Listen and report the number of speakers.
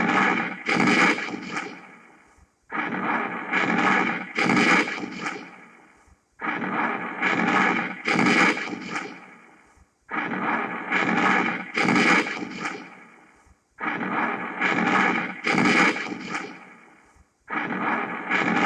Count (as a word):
zero